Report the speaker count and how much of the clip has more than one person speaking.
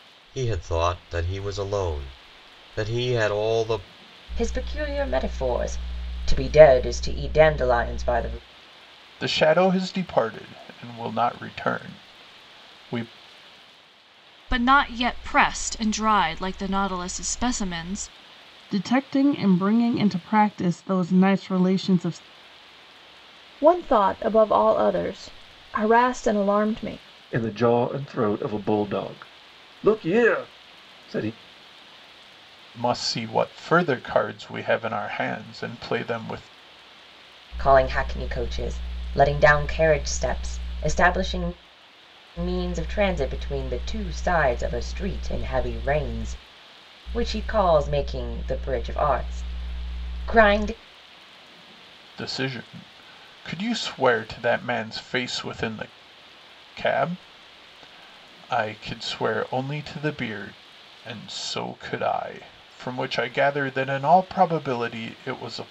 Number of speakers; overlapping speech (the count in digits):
7, no overlap